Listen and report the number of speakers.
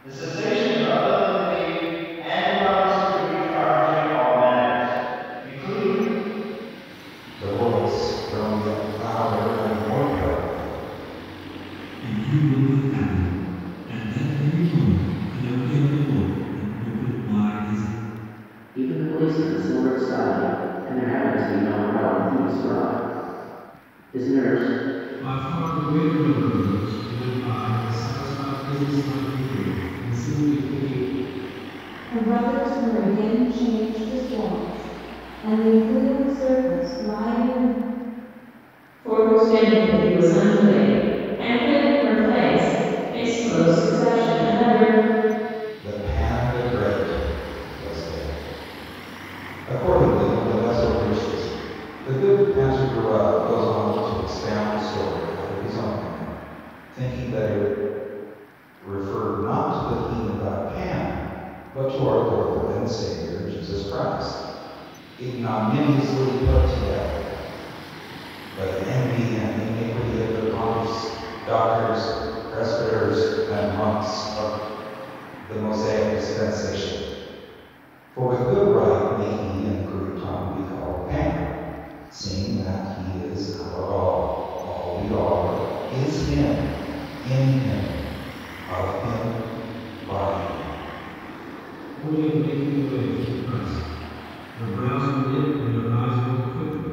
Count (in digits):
7